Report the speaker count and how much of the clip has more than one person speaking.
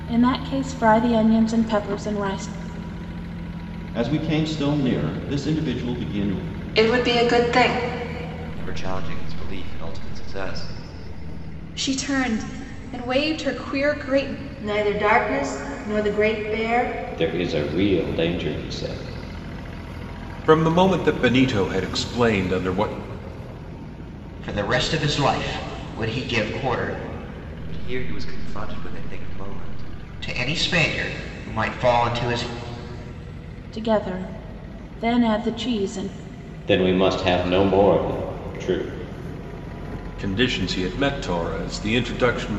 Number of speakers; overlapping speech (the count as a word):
nine, no overlap